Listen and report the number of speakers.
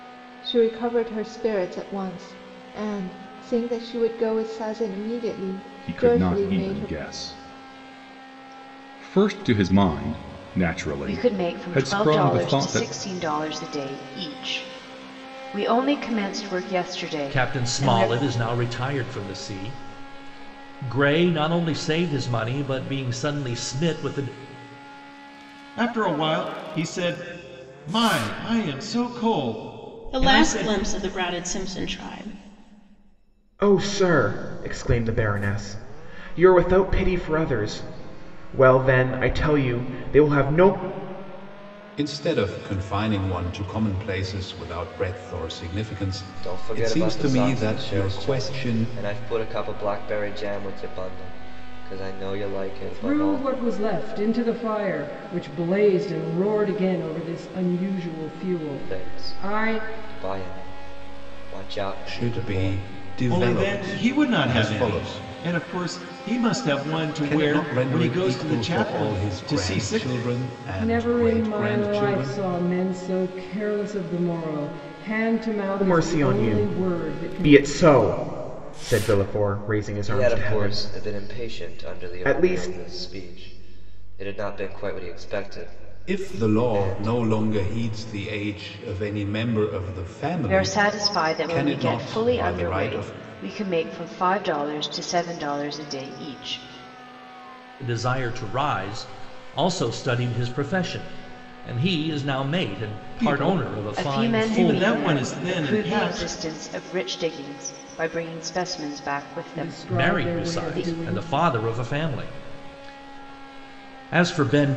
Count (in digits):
10